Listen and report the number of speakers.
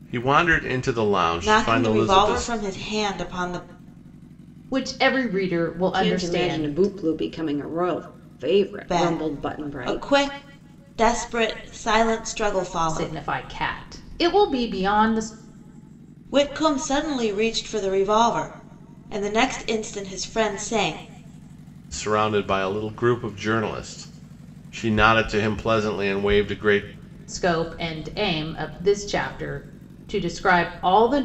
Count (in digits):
4